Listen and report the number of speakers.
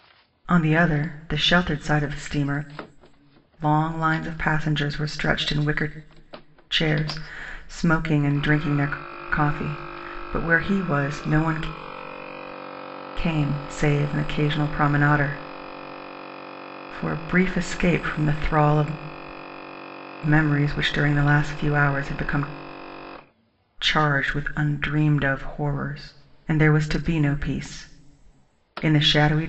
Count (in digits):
1